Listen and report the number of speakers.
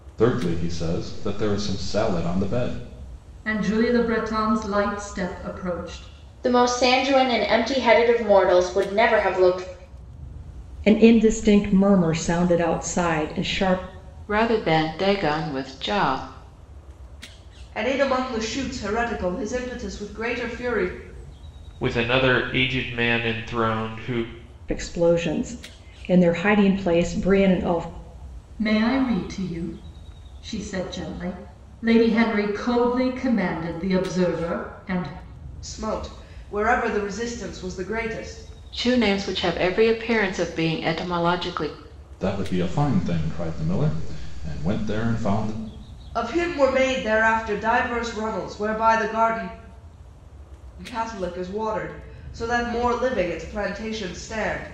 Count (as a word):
seven